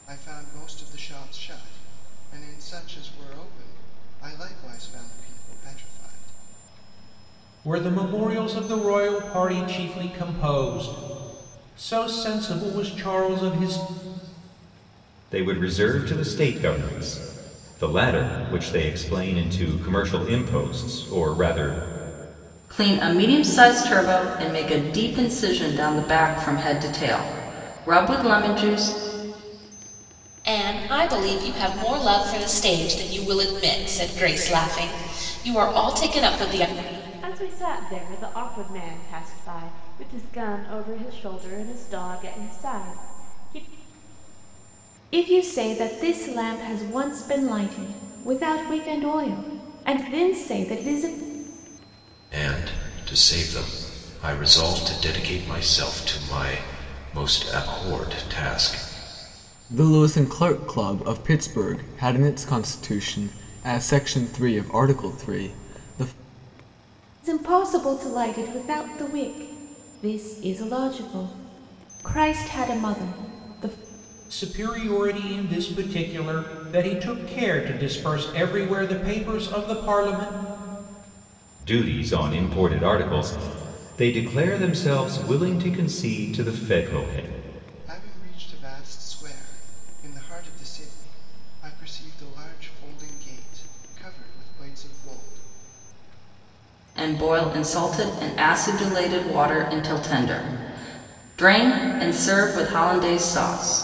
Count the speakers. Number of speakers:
9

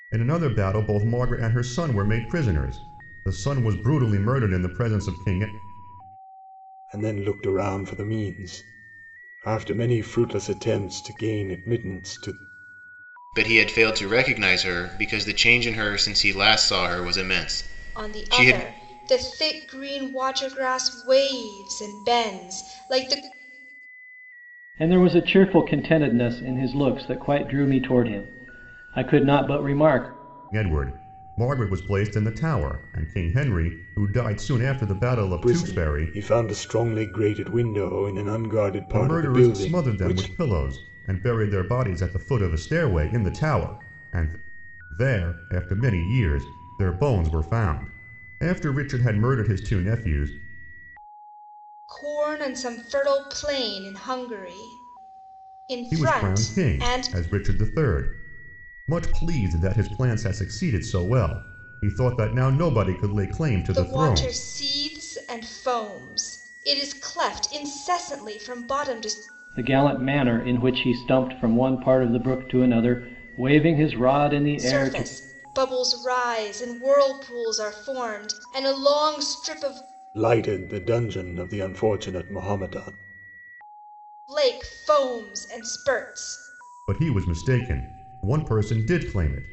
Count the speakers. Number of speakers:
5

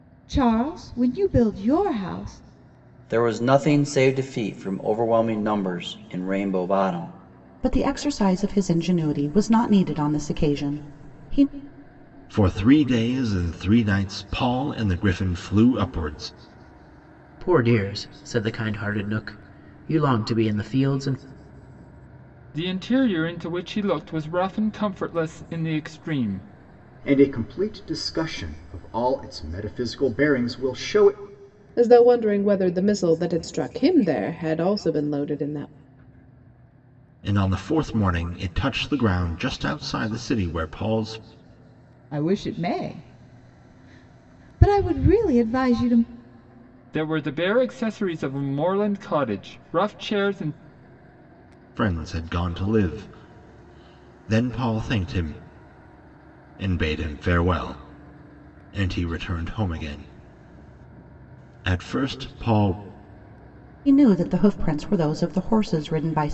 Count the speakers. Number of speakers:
8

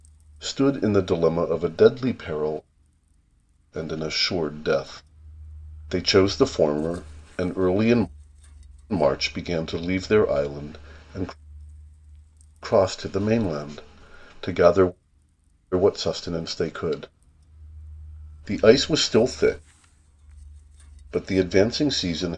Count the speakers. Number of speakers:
1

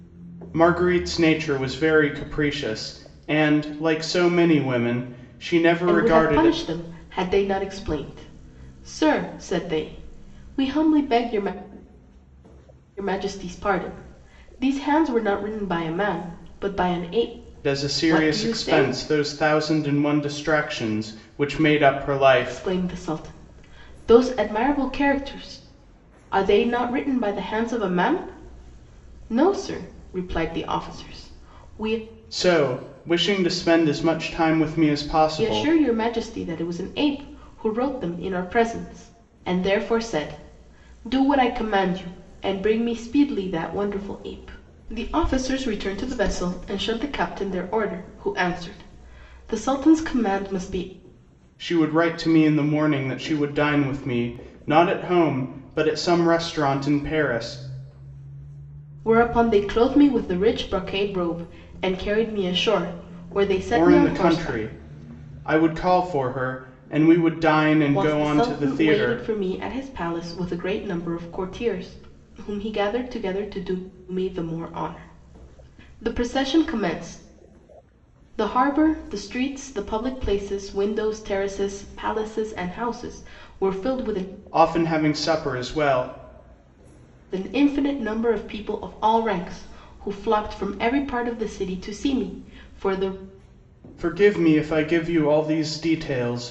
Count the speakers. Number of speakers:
2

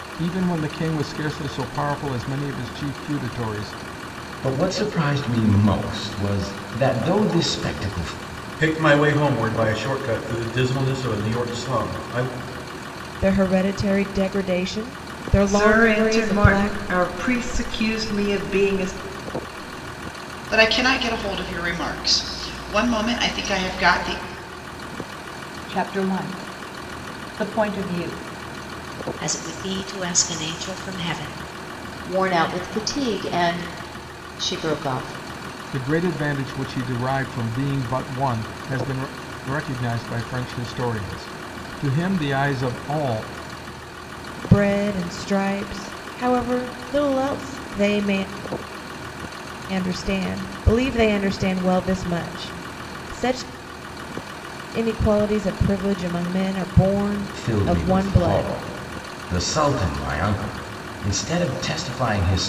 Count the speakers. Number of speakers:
9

